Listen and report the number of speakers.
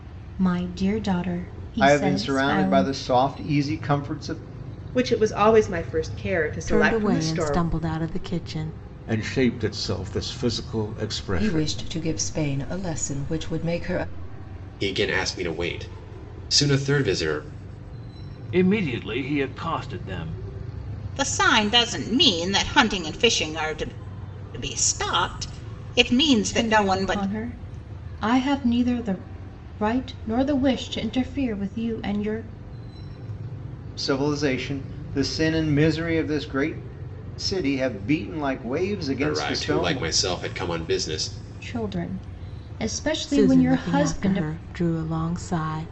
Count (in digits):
9